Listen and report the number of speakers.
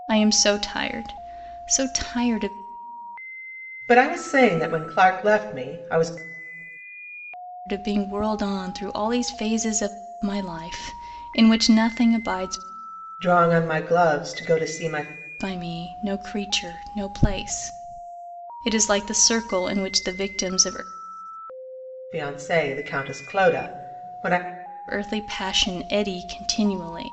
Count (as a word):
two